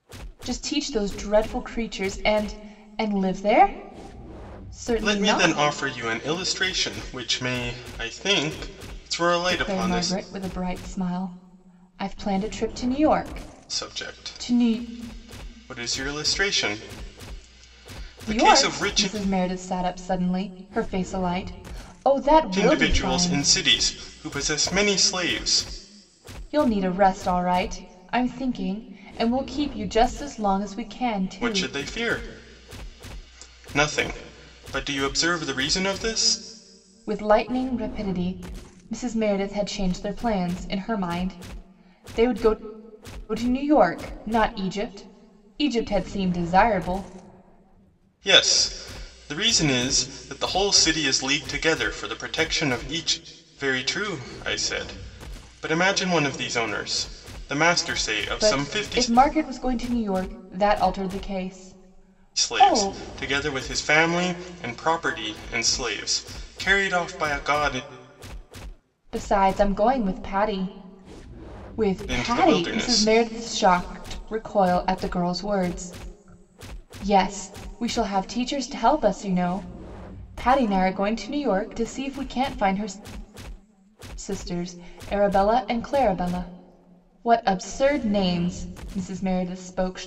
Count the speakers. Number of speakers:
2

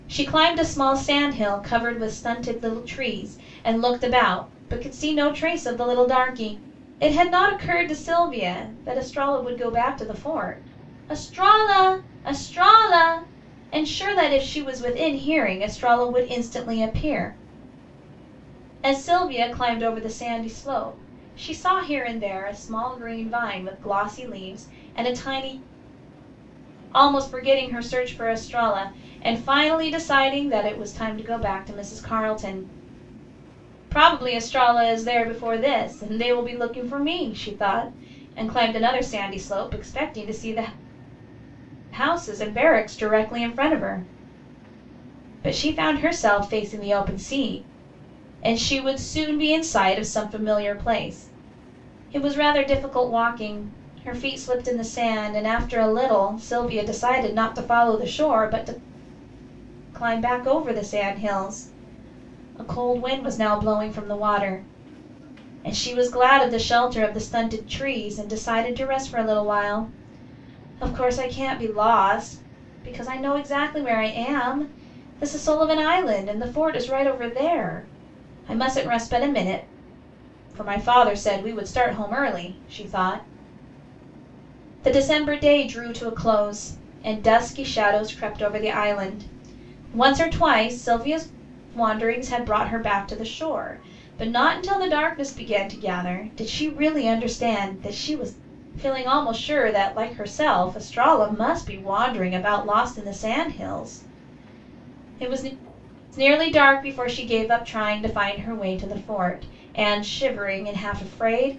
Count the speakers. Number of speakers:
1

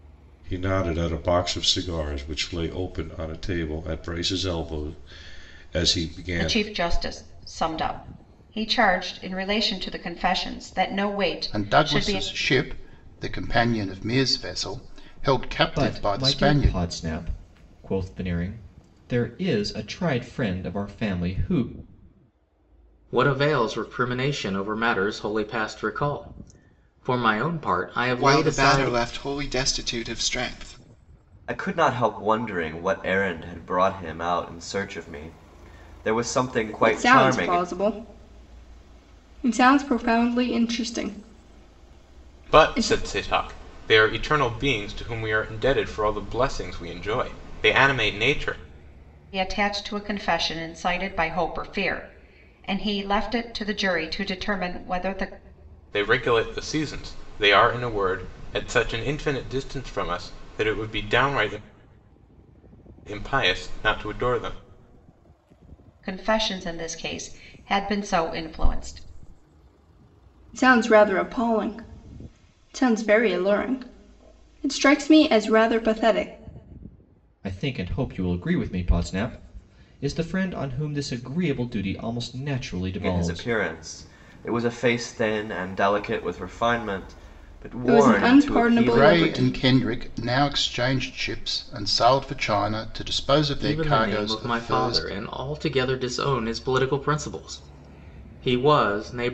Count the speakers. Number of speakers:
9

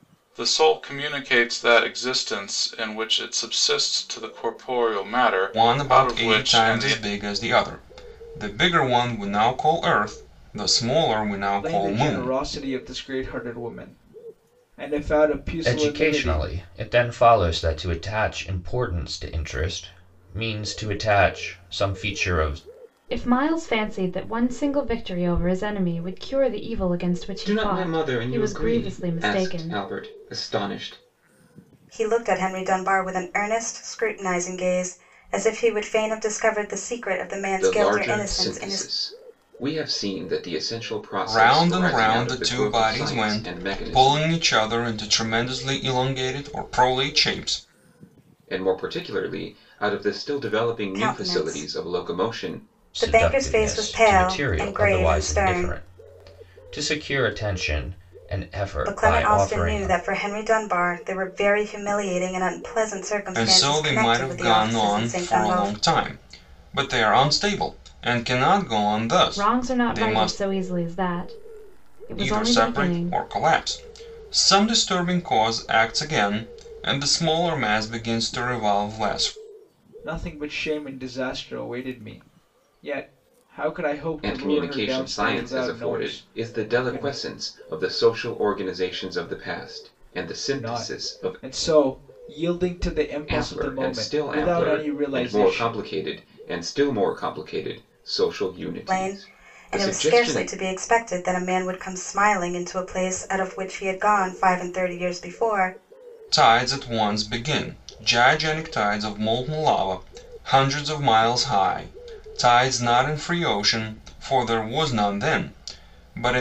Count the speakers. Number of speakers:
7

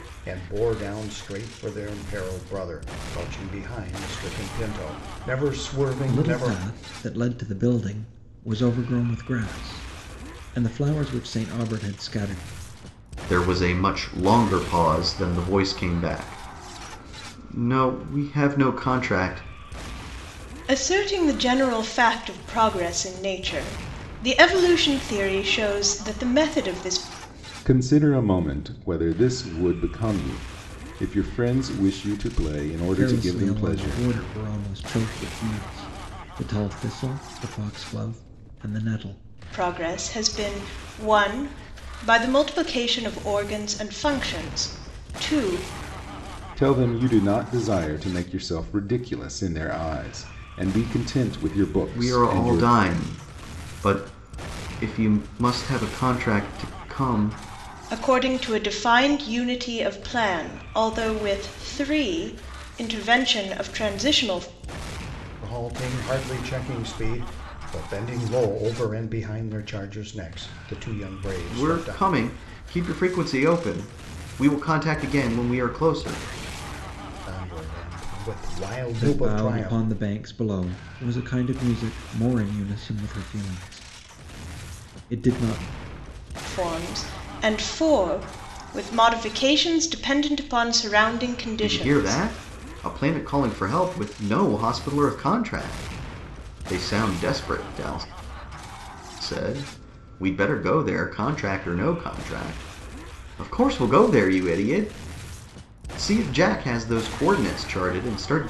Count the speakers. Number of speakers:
5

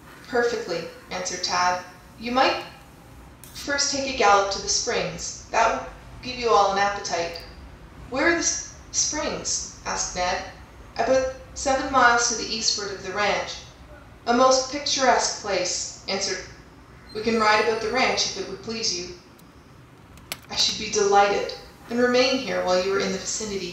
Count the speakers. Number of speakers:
1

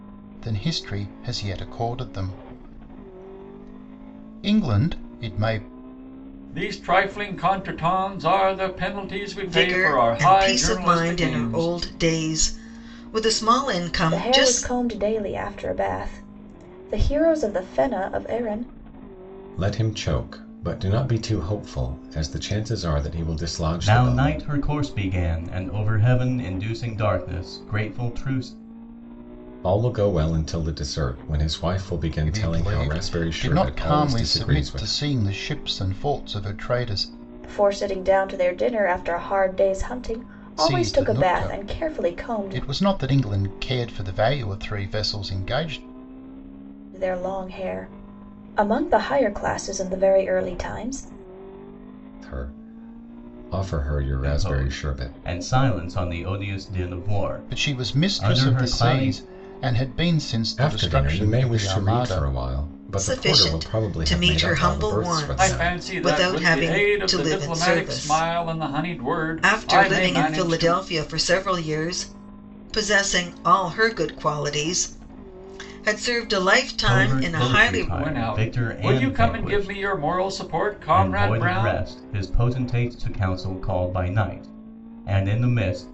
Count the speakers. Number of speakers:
6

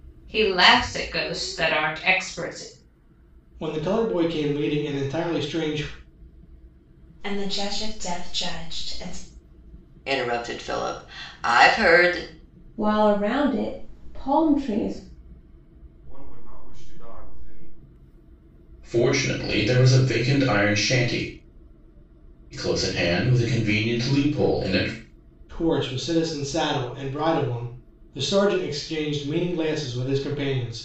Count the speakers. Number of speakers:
7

